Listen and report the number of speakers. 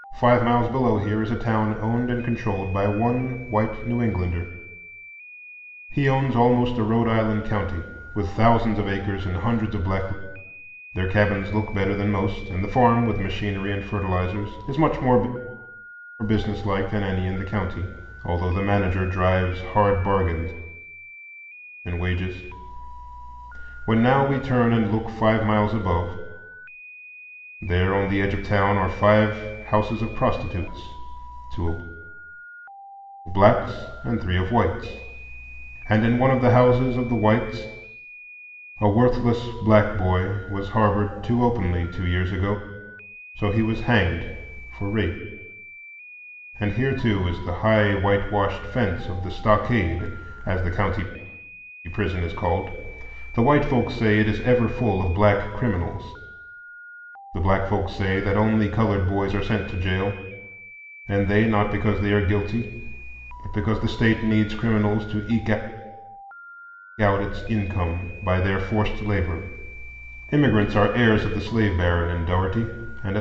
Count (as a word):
one